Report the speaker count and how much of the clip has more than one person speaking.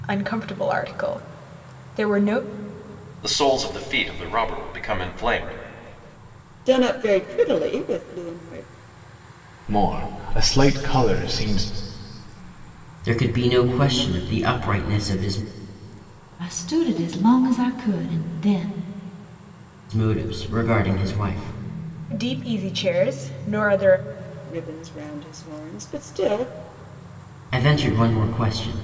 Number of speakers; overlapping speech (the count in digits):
6, no overlap